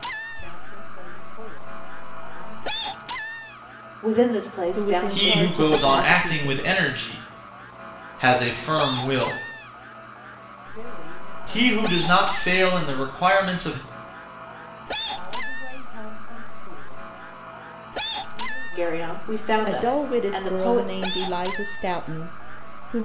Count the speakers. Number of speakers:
4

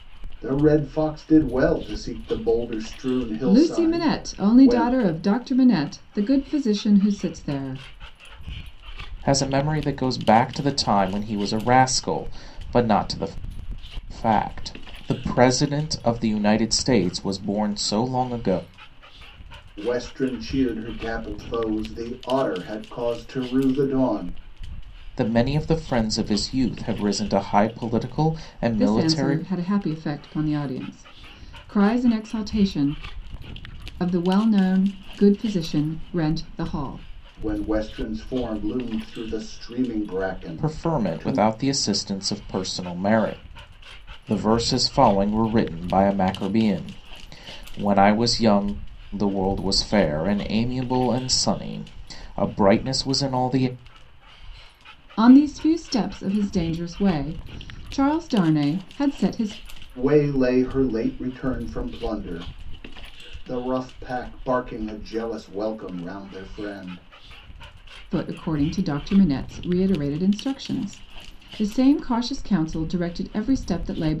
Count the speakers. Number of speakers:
3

